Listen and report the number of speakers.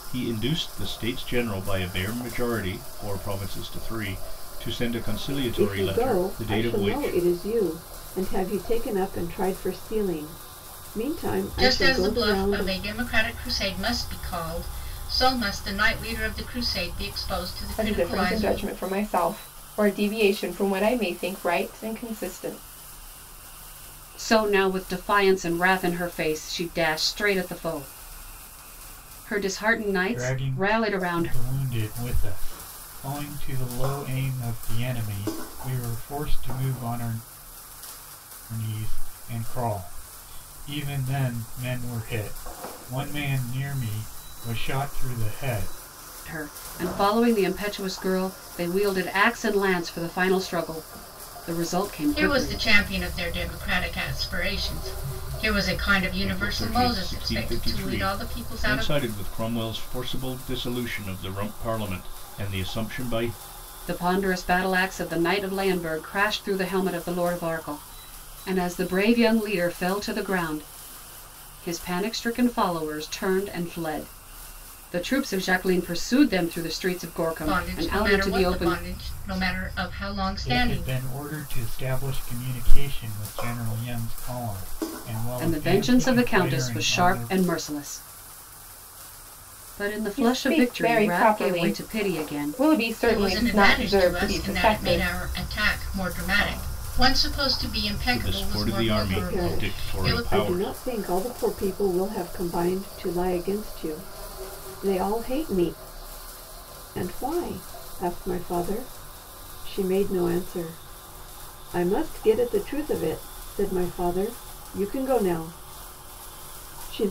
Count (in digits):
6